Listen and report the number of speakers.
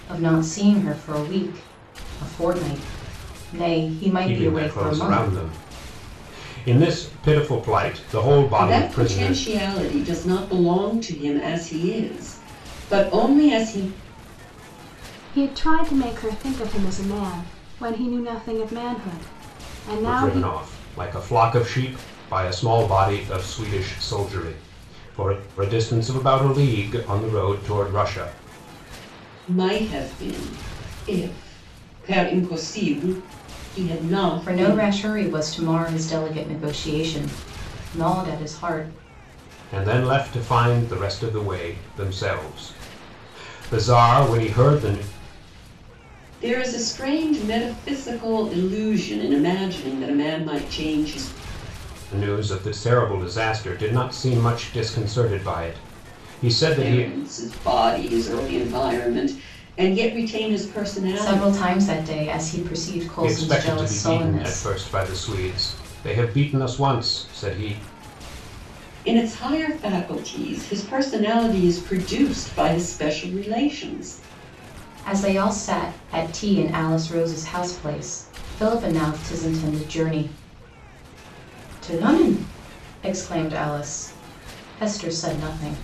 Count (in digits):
4